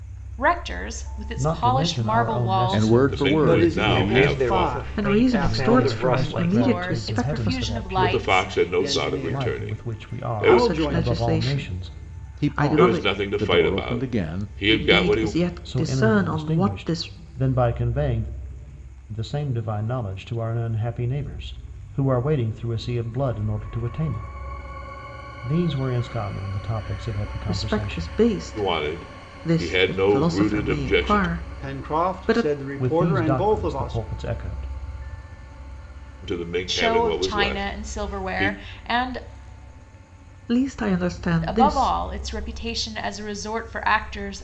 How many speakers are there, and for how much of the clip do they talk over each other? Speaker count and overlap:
seven, about 52%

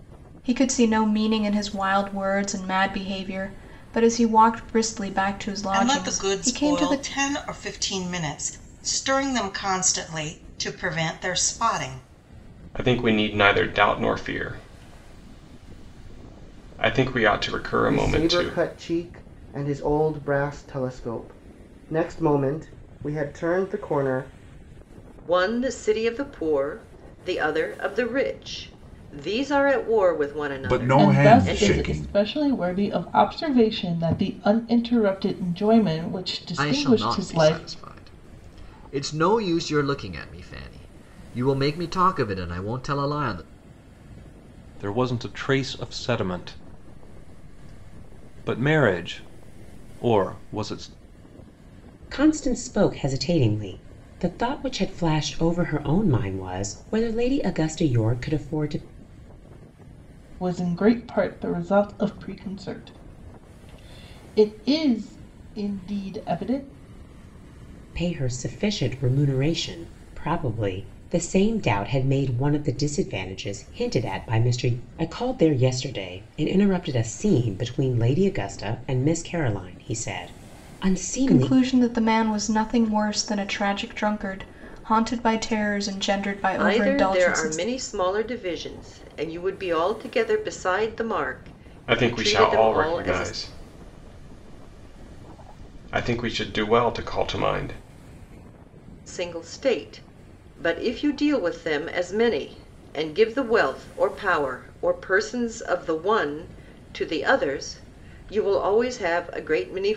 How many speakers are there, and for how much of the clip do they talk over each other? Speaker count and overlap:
ten, about 7%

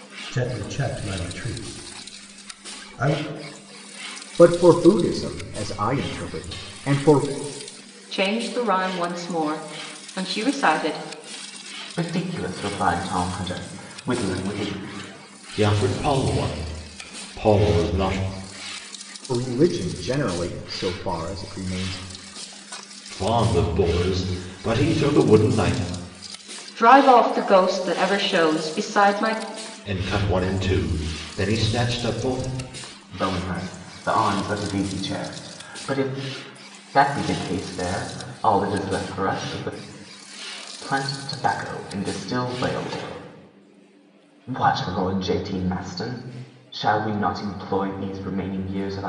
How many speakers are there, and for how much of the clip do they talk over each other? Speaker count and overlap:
five, no overlap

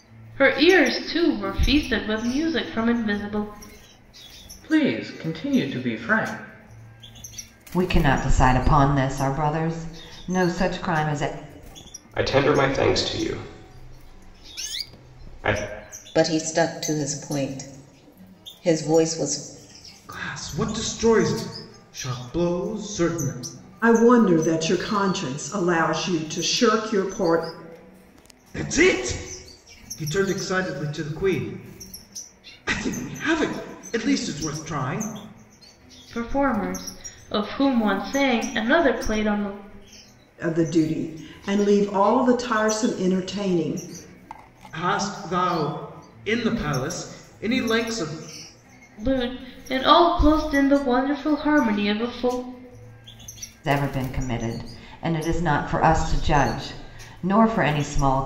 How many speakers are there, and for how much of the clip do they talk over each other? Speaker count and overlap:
seven, no overlap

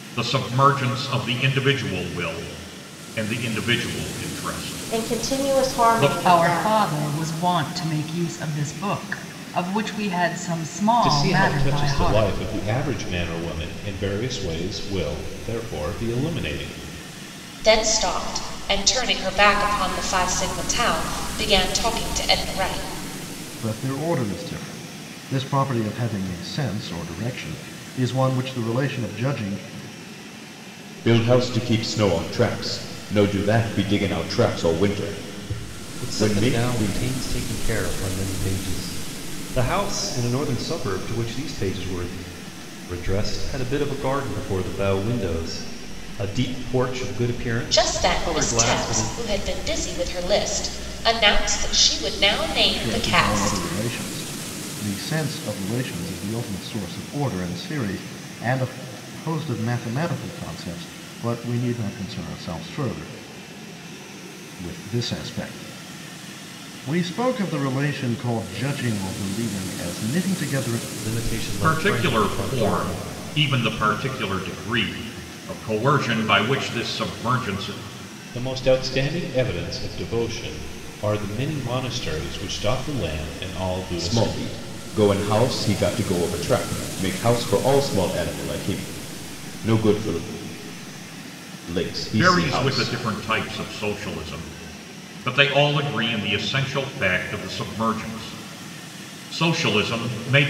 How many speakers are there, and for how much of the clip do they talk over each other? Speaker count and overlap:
eight, about 9%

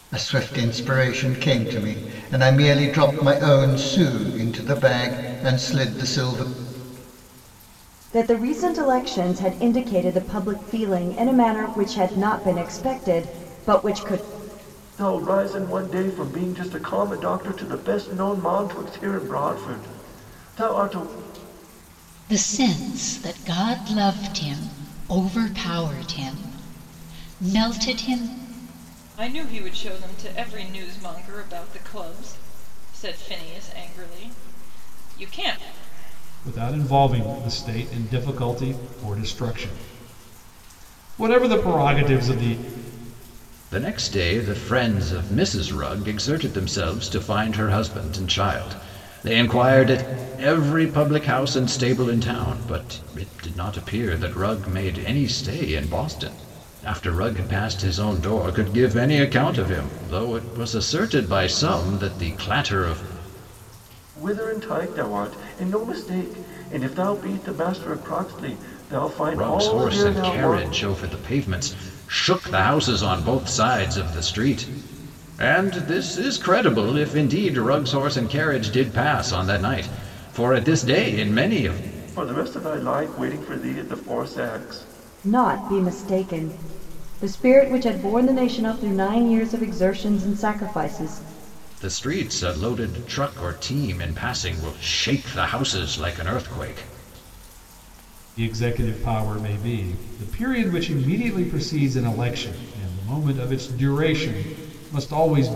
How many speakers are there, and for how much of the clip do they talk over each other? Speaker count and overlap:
seven, about 1%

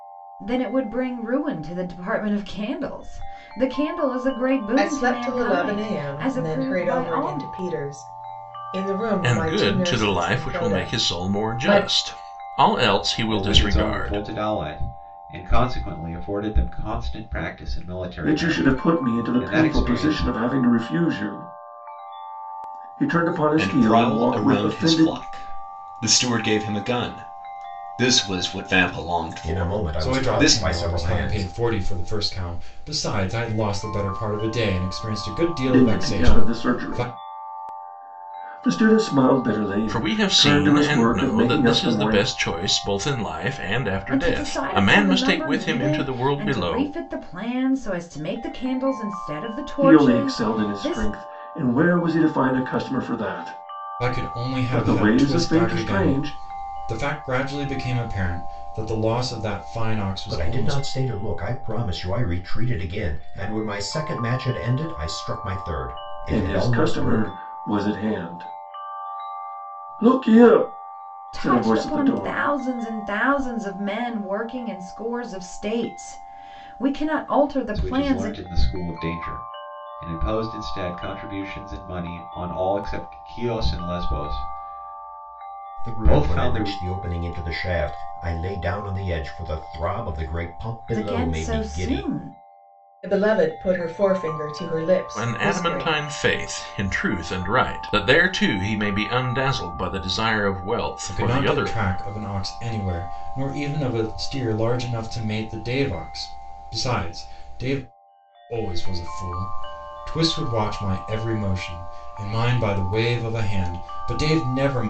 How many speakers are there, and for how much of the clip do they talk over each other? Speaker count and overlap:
eight, about 26%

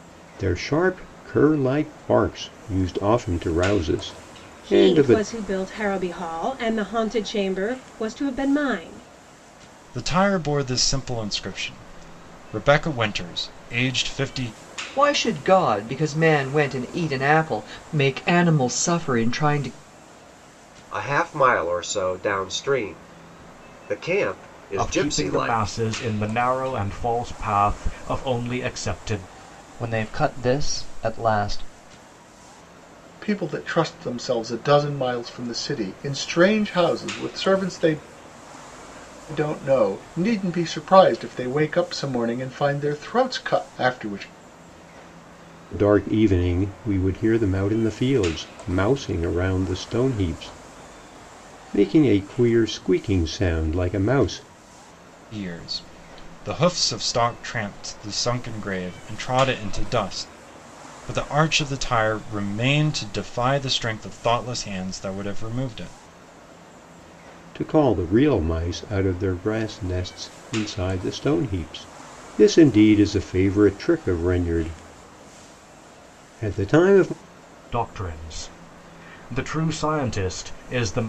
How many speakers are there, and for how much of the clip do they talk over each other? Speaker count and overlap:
eight, about 2%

